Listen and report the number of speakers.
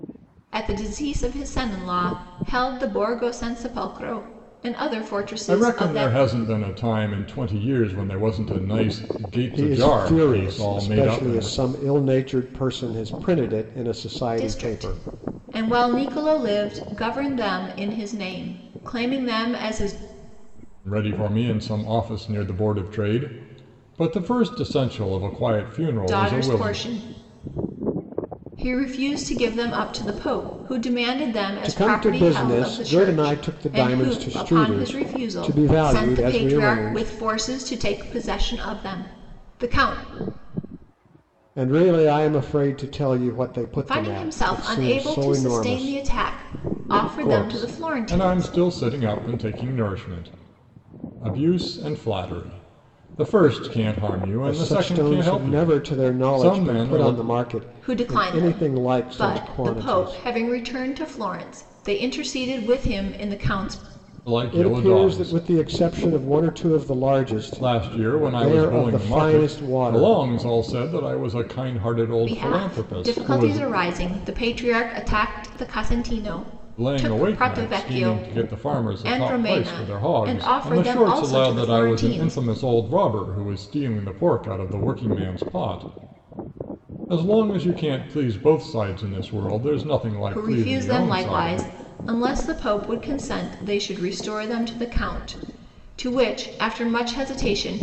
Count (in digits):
3